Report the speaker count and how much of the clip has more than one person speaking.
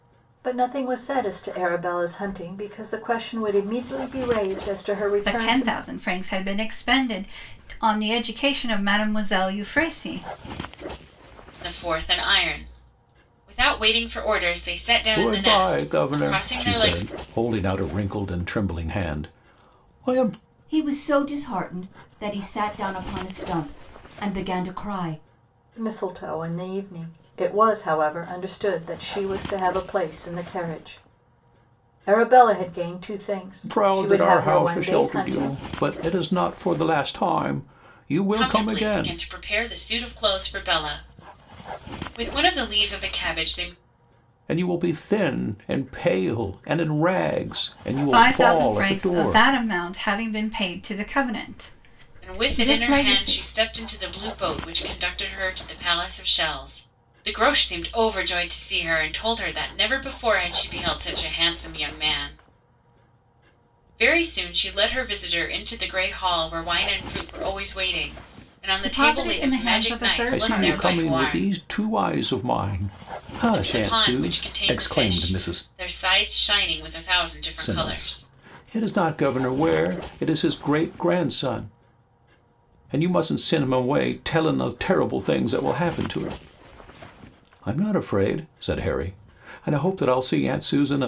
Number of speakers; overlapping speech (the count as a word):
five, about 15%